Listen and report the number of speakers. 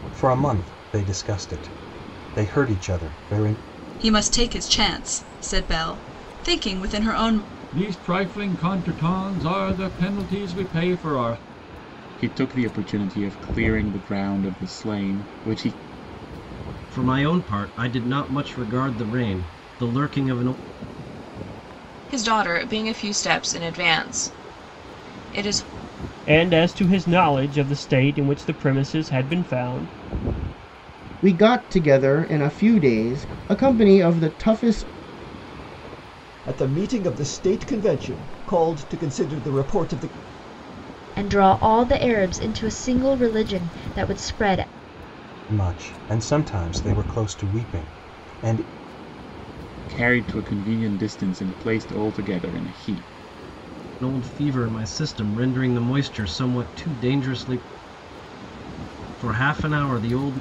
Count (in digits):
10